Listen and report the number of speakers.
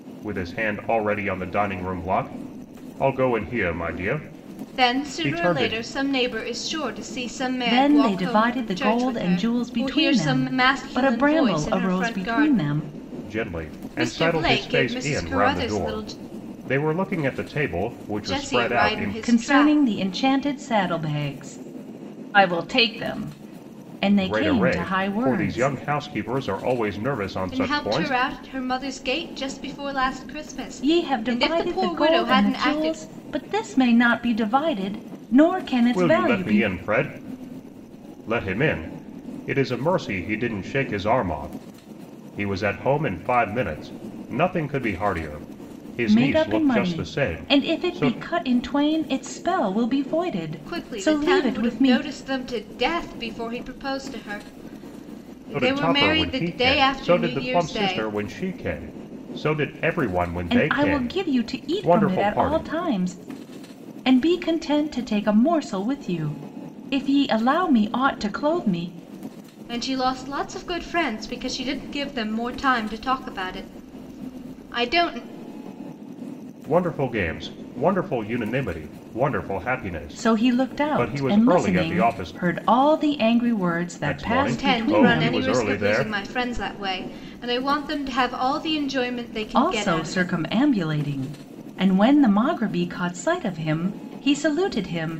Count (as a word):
three